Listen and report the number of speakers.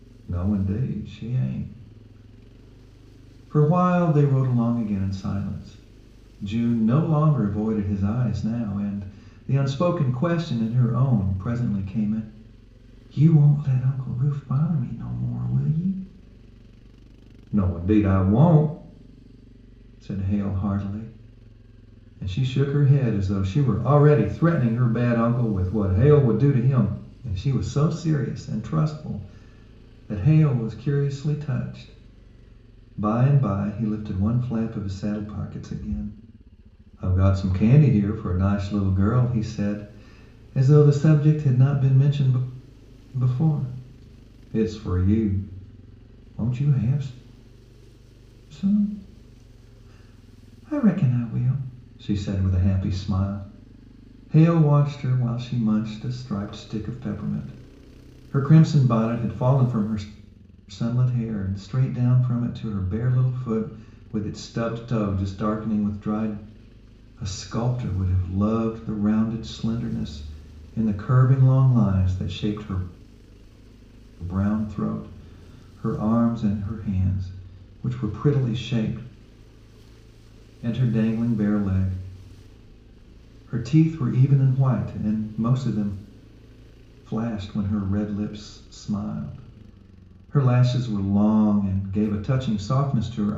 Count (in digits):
1